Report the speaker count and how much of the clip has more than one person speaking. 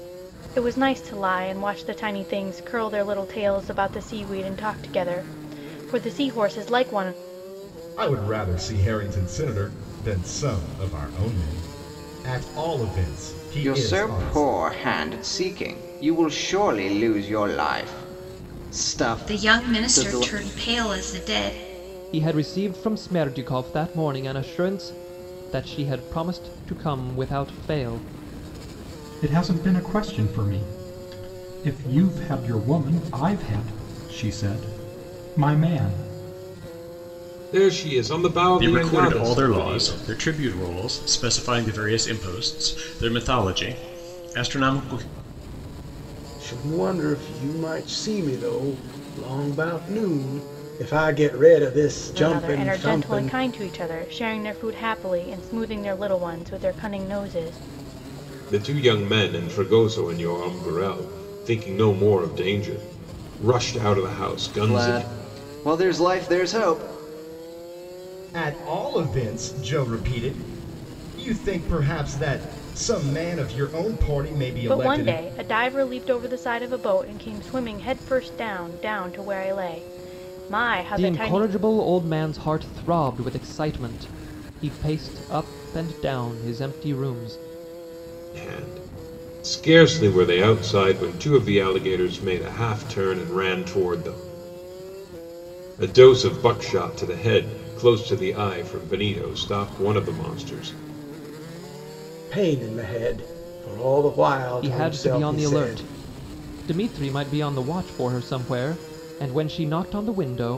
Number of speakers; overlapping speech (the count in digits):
9, about 7%